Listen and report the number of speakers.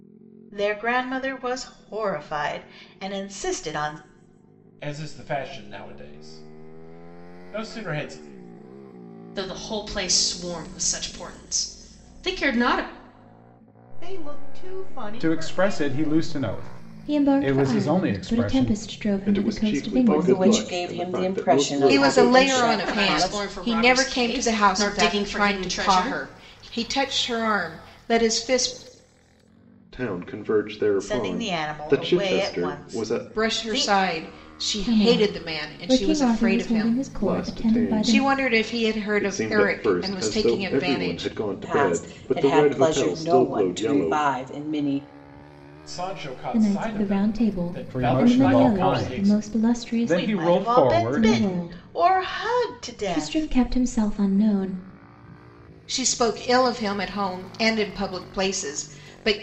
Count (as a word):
nine